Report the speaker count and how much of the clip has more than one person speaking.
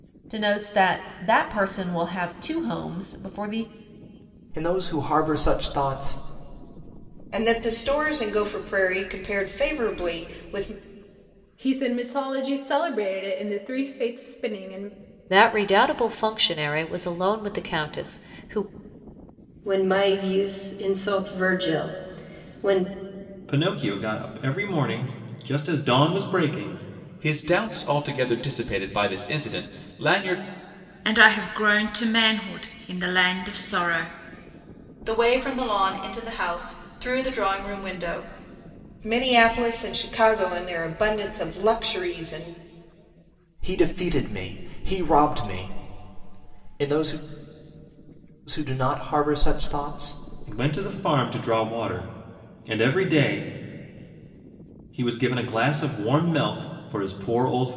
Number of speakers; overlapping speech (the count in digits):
10, no overlap